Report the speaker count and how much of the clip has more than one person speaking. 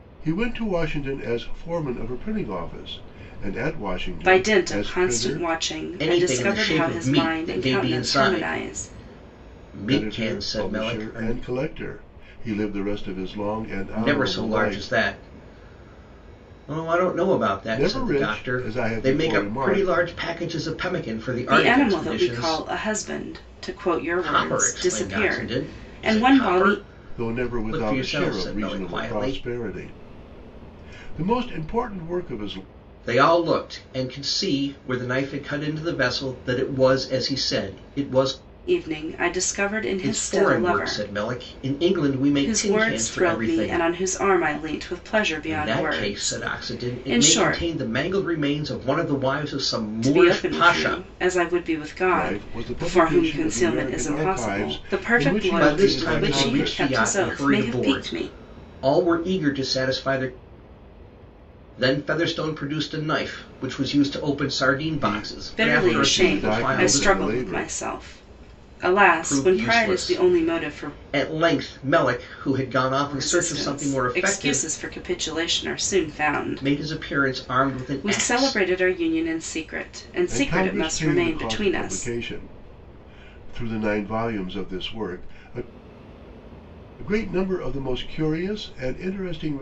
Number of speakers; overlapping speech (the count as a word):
three, about 42%